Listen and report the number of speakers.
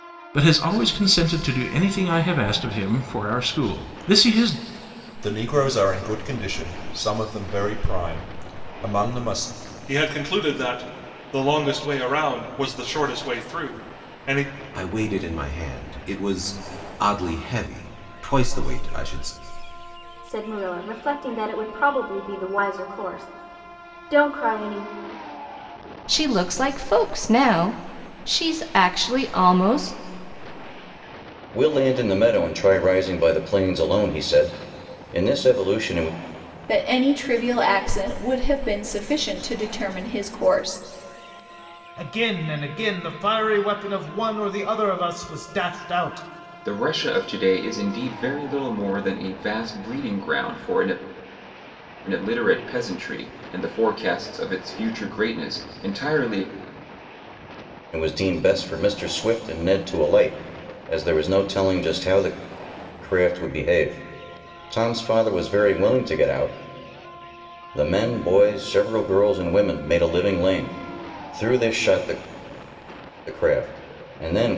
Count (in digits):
10